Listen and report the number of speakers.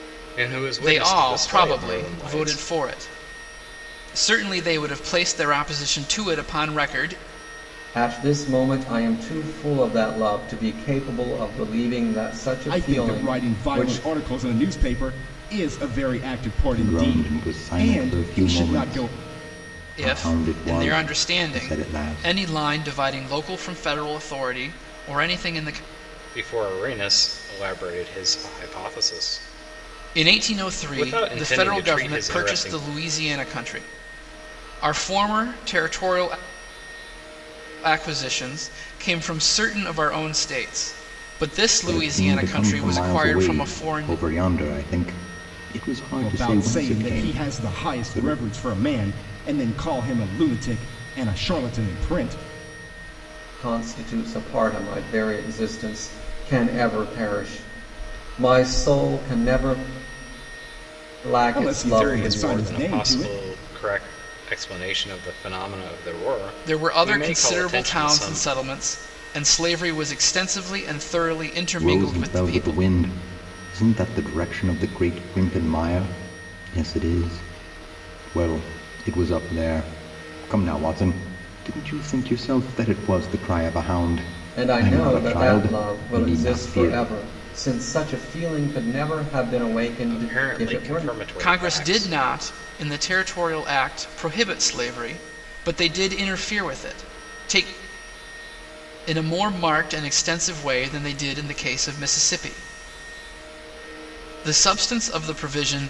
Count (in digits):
5